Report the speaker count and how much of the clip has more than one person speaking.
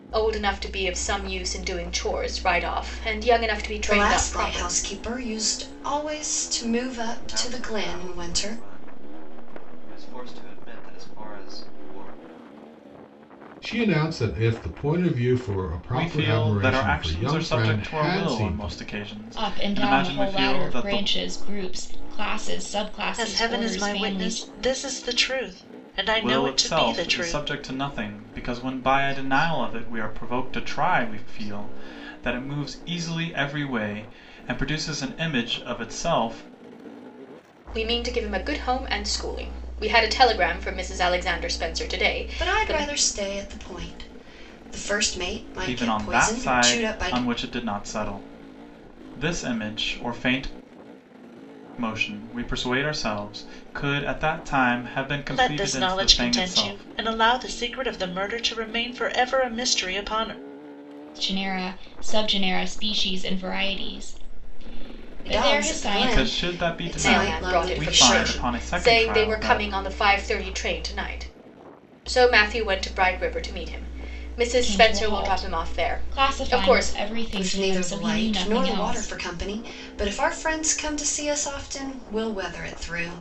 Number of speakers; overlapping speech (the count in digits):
7, about 30%